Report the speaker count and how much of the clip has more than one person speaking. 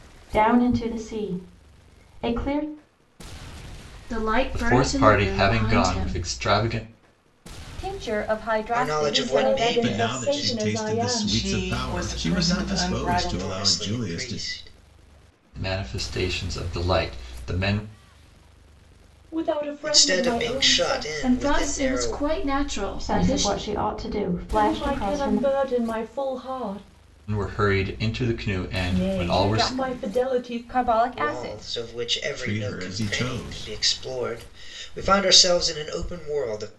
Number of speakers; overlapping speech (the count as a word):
eight, about 41%